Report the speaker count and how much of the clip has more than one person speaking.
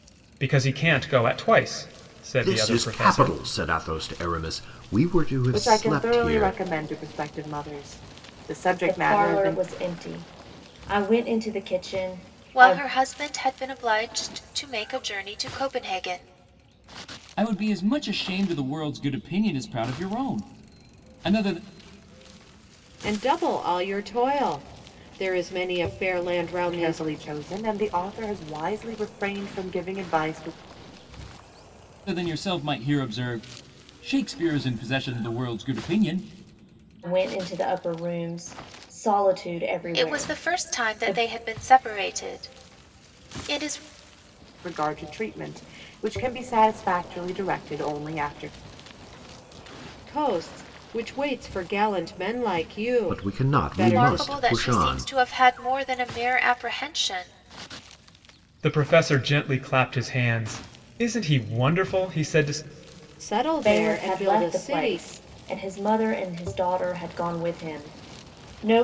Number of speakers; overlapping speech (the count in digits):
7, about 12%